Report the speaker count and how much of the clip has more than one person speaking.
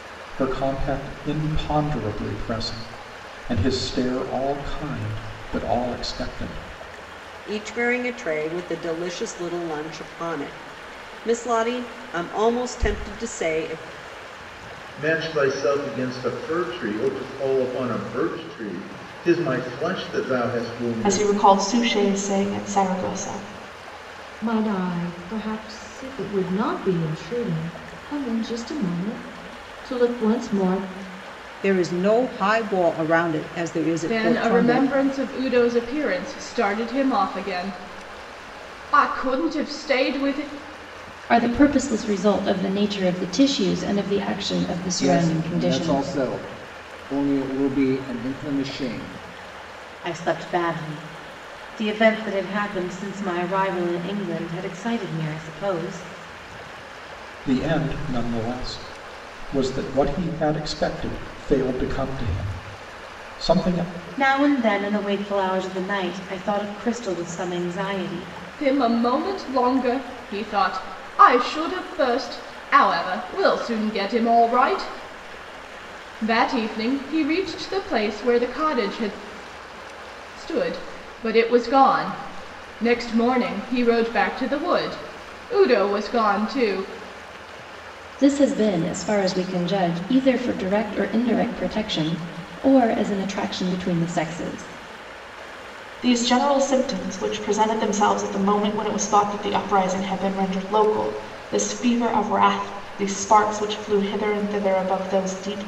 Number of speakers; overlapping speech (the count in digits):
10, about 2%